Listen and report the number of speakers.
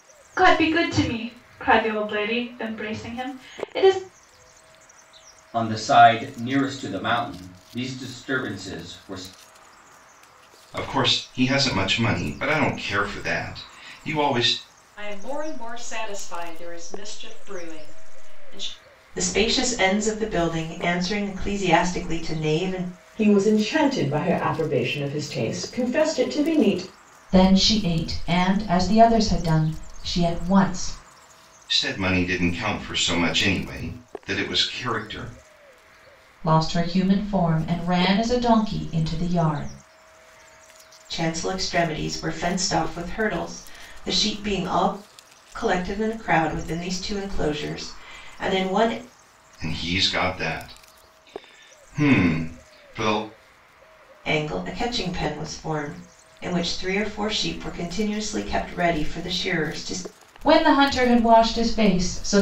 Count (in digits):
7